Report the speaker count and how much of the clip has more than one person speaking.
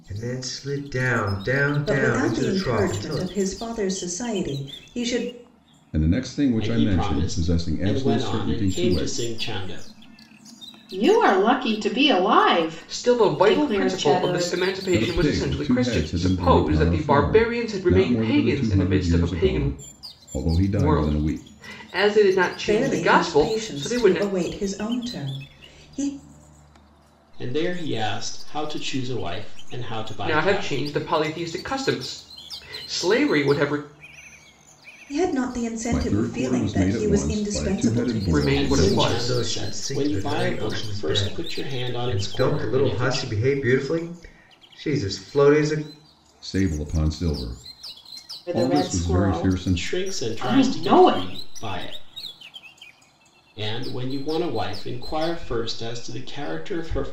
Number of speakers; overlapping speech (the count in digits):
6, about 42%